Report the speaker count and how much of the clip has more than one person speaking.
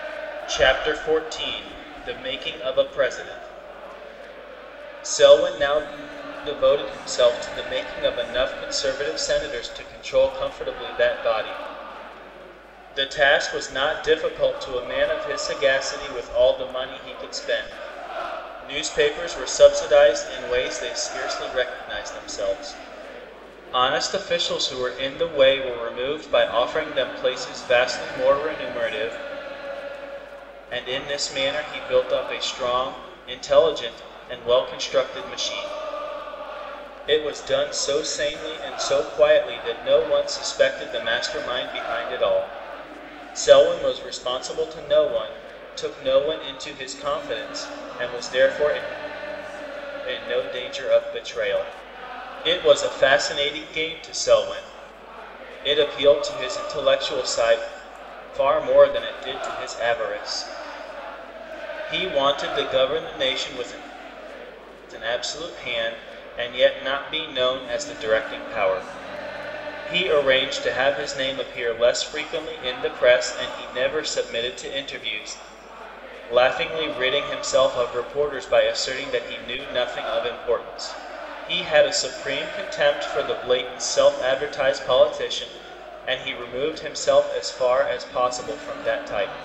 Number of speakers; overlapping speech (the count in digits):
1, no overlap